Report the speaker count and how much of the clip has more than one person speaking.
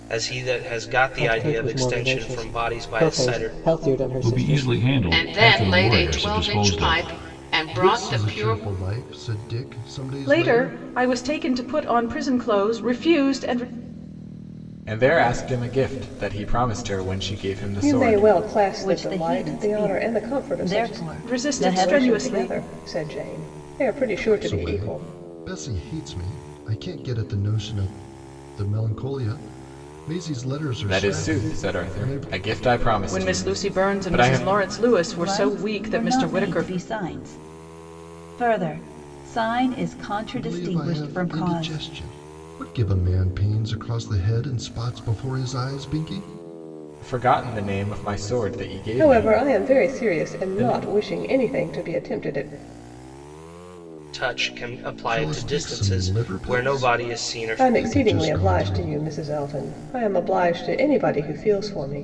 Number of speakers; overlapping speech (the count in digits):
9, about 37%